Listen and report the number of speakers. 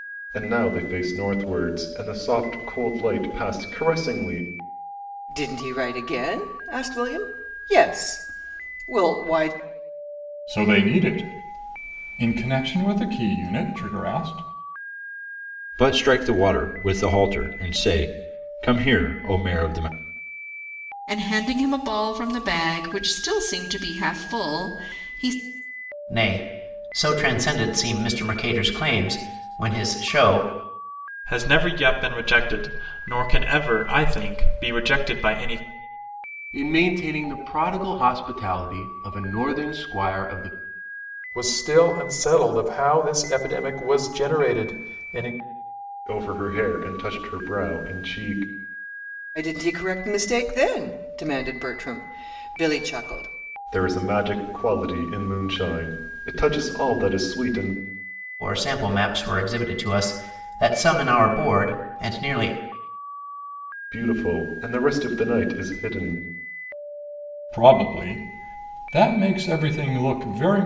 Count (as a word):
nine